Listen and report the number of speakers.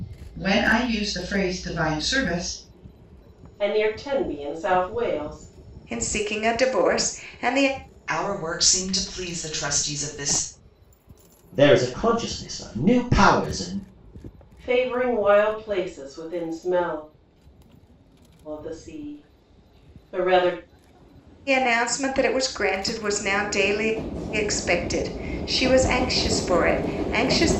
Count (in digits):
5